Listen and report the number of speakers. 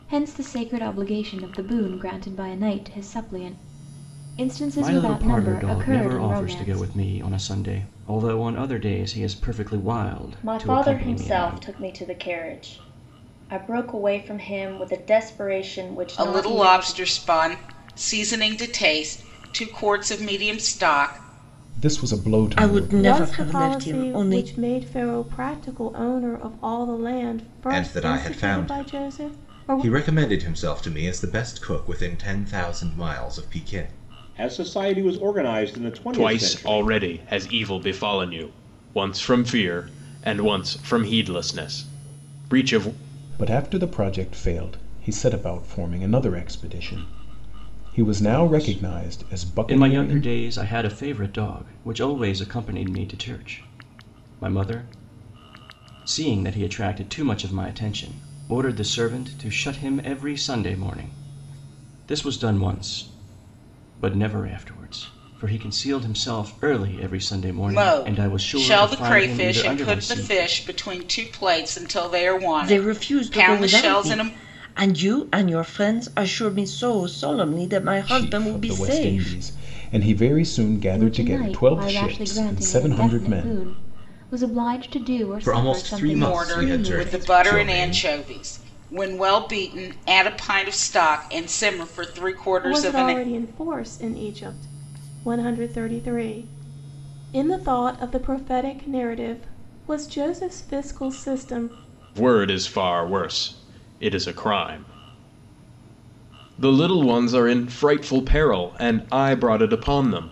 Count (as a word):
ten